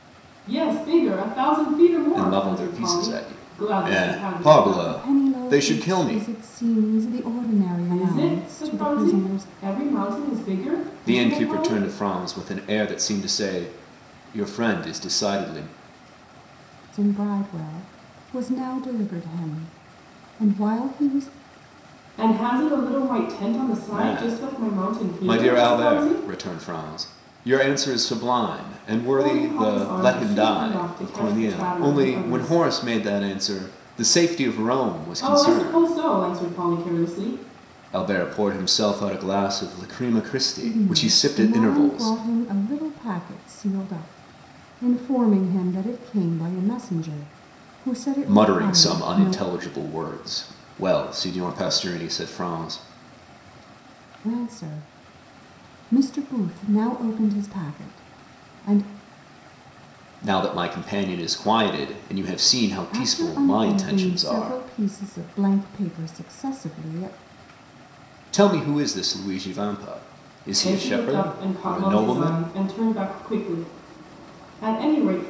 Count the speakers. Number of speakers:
3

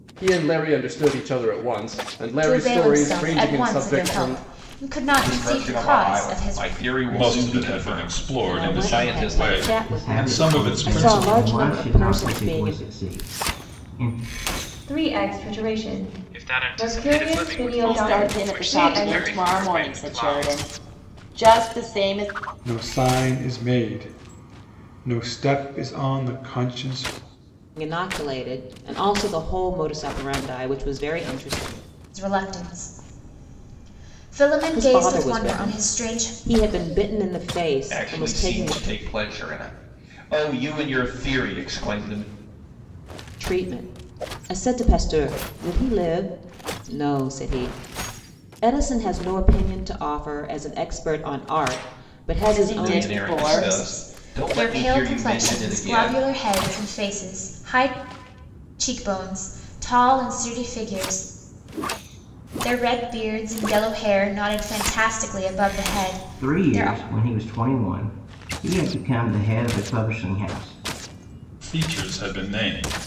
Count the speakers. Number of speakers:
10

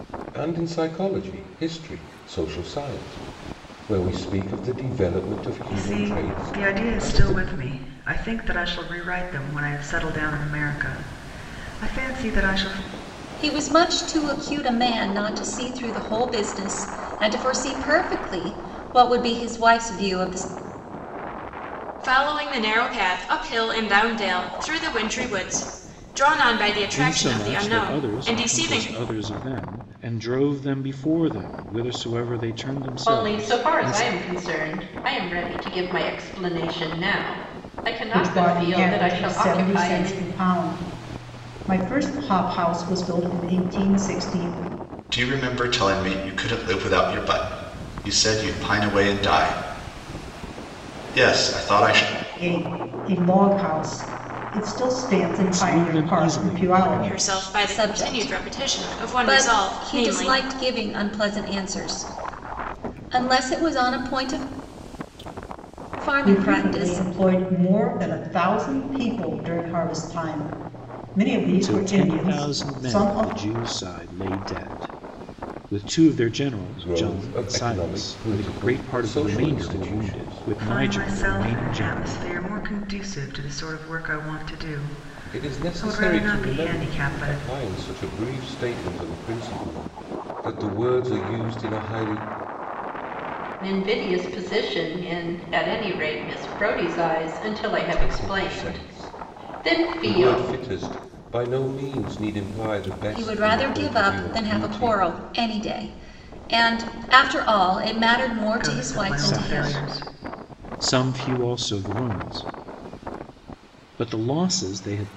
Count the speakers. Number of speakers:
8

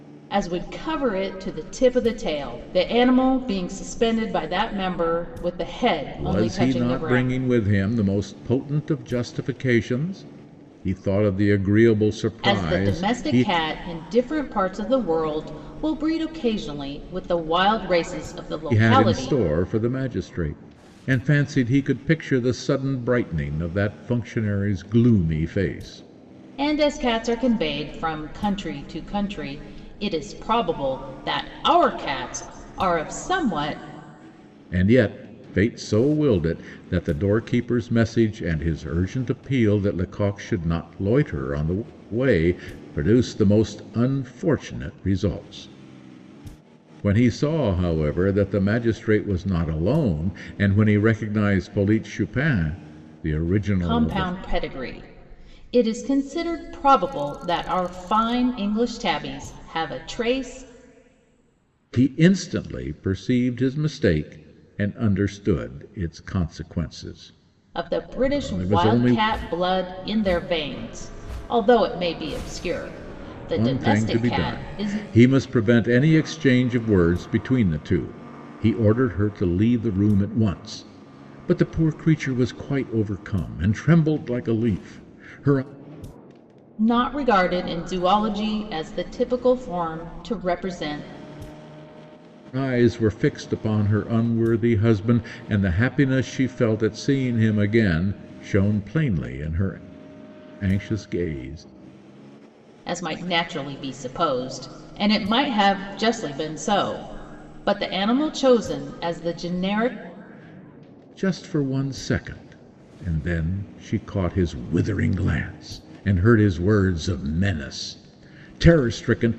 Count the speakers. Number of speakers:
2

